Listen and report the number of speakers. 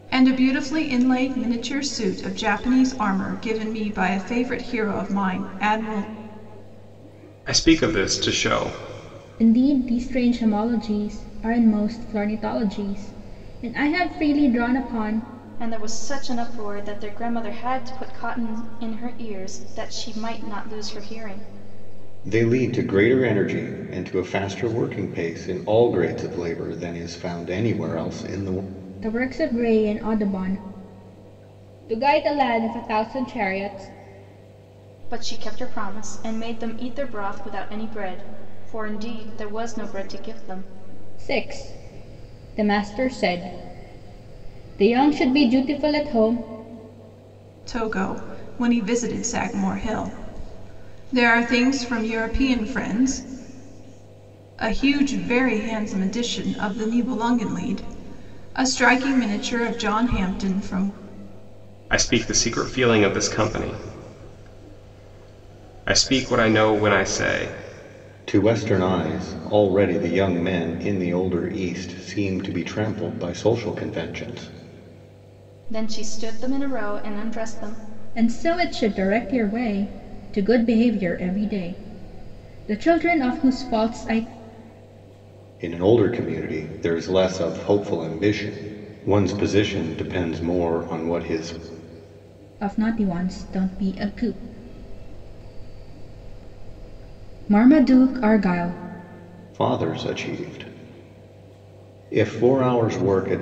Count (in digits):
5